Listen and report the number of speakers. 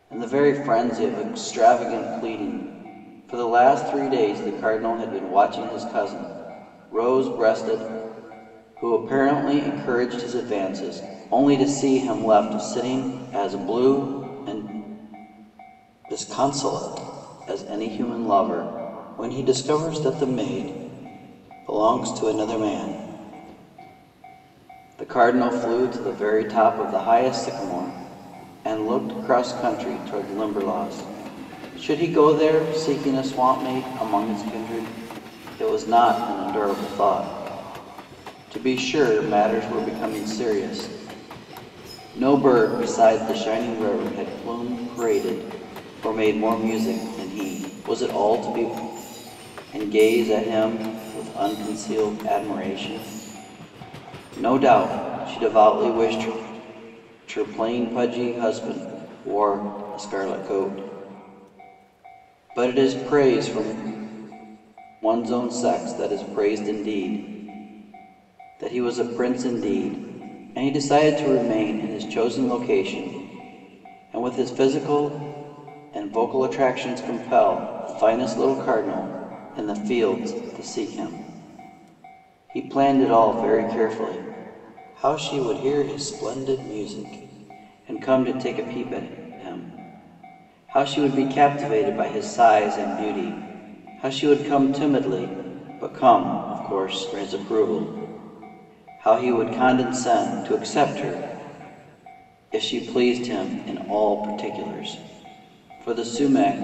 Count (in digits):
1